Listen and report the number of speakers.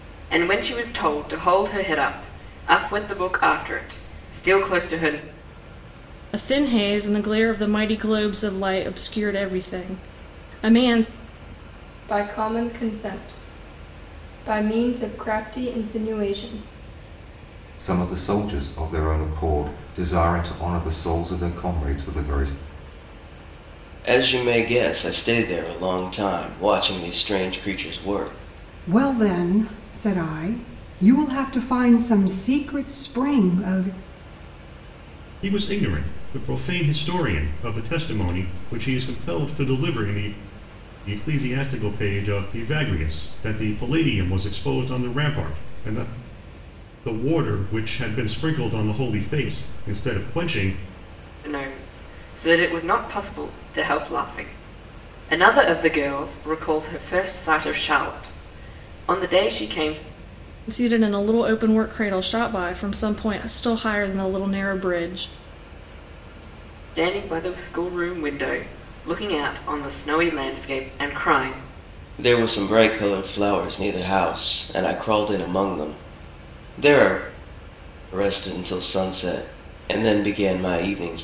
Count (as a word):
seven